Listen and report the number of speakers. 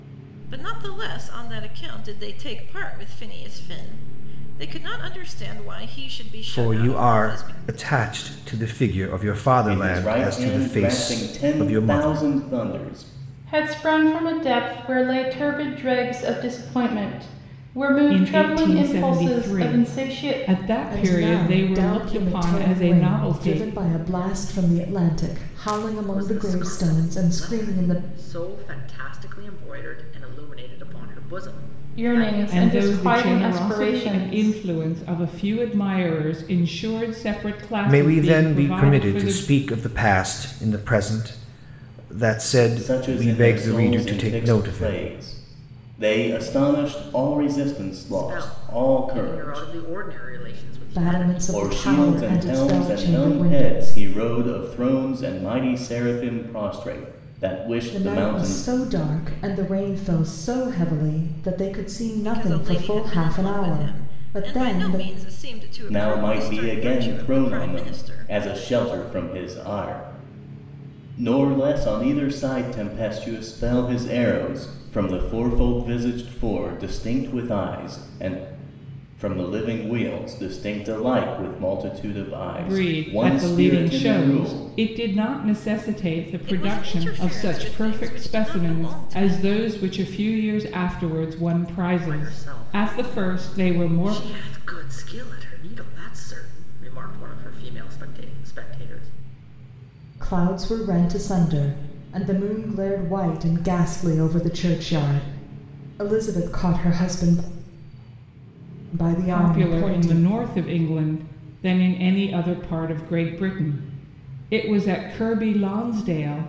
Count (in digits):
7